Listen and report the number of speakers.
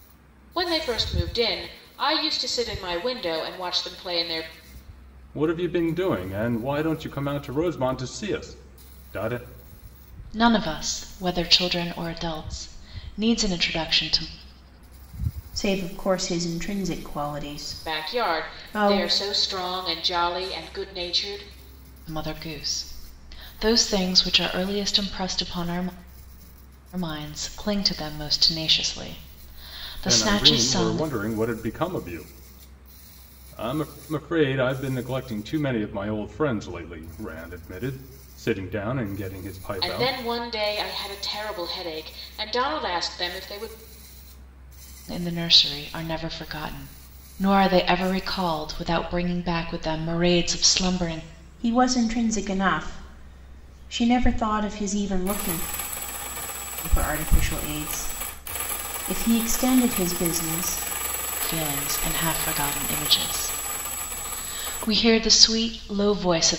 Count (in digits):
4